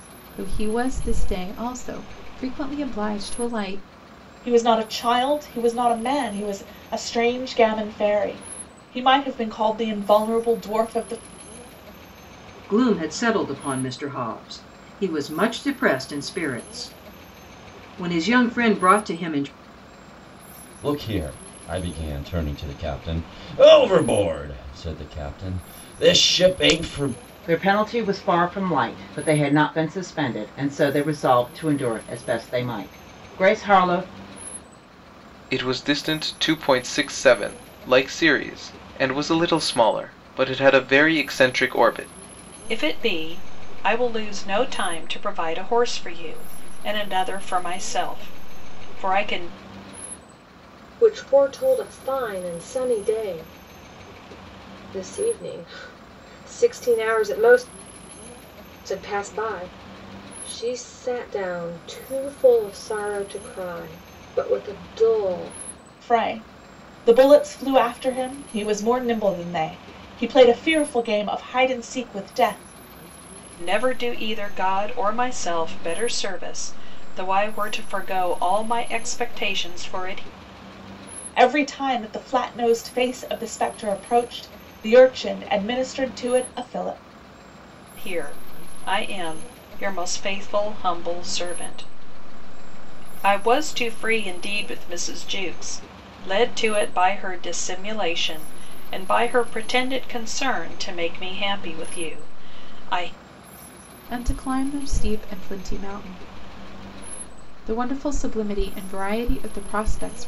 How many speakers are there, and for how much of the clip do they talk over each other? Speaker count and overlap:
eight, no overlap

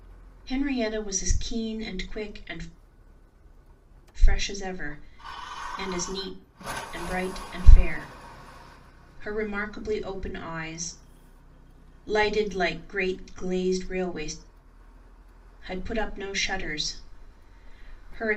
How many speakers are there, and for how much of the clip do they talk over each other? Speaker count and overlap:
one, no overlap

